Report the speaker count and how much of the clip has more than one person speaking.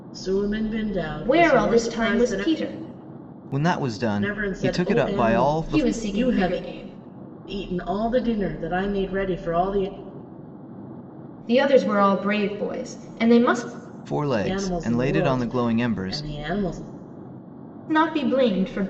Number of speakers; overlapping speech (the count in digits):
3, about 29%